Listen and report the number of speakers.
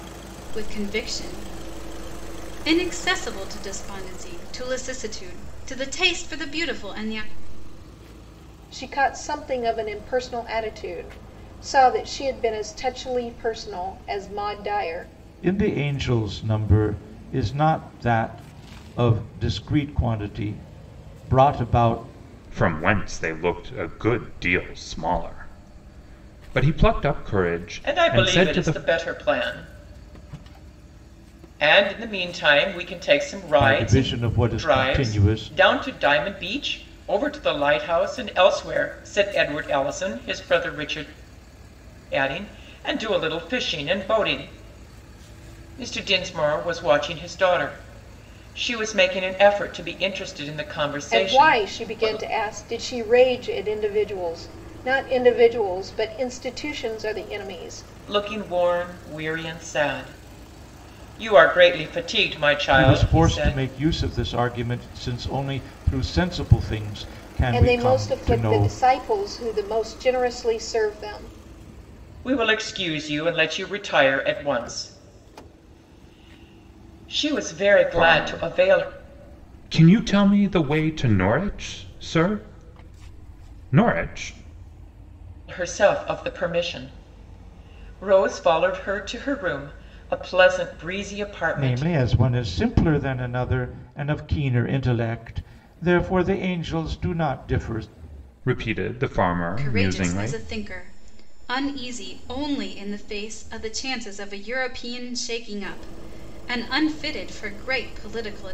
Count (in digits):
5